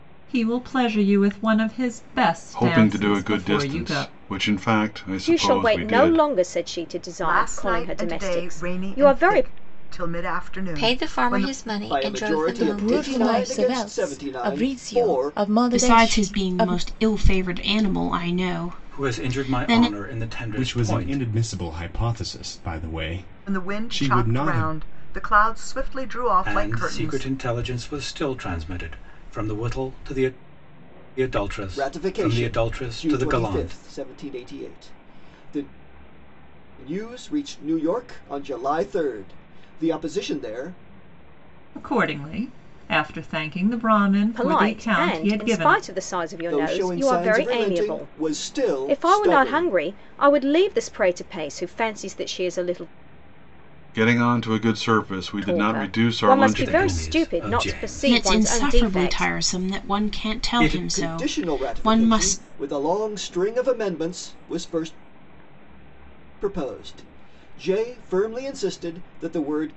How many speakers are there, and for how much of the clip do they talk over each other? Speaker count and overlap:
ten, about 39%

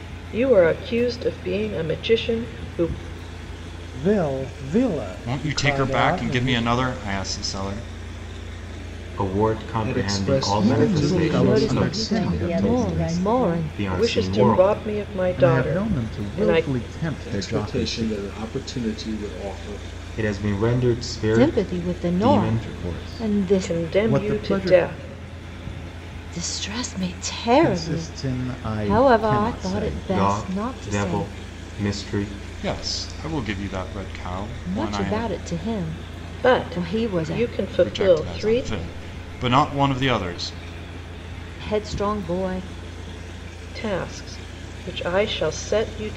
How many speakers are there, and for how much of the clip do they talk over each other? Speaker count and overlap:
eight, about 39%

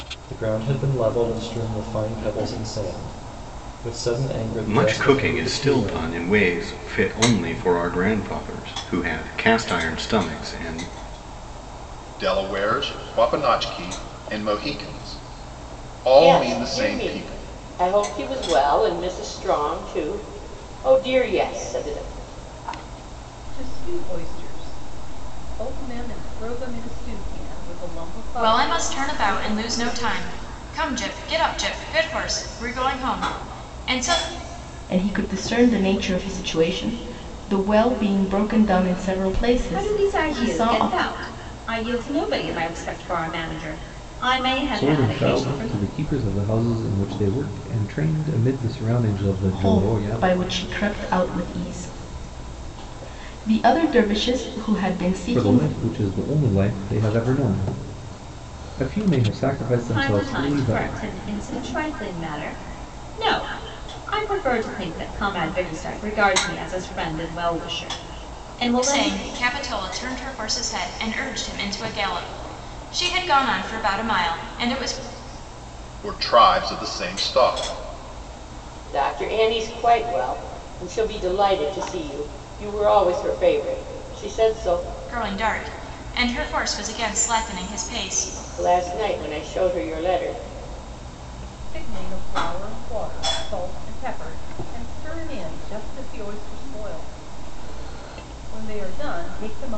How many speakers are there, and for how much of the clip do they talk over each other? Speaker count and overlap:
nine, about 9%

